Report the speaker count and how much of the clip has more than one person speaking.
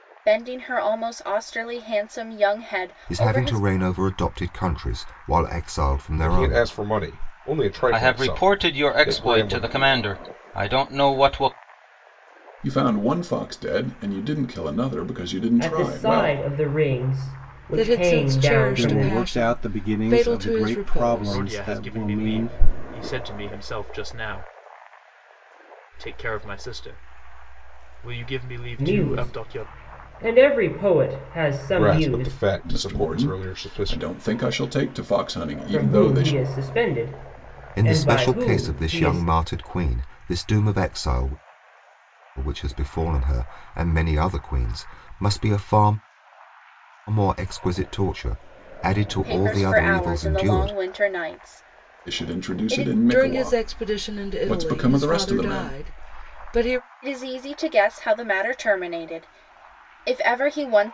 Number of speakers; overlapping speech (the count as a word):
nine, about 32%